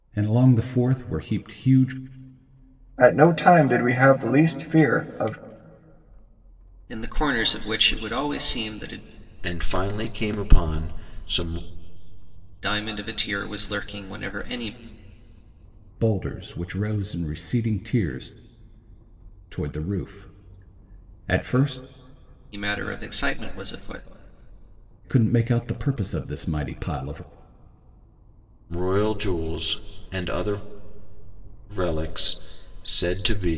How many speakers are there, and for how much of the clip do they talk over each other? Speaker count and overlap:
4, no overlap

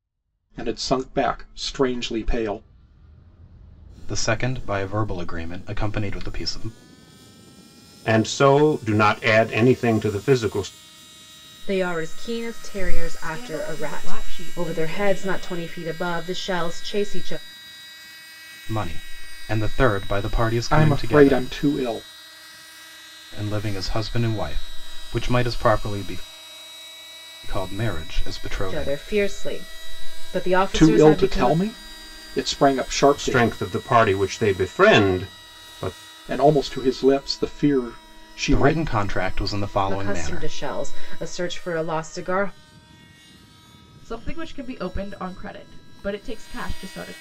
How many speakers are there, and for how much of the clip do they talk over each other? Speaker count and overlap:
5, about 12%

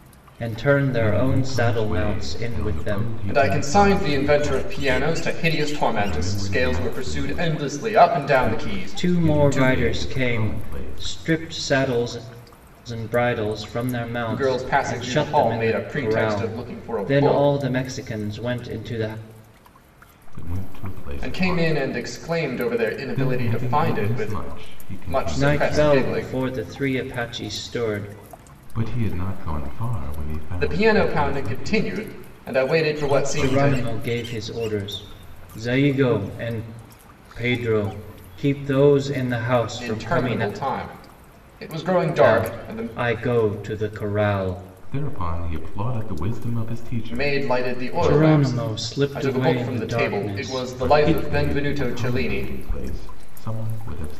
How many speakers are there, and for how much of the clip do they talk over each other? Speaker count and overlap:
3, about 46%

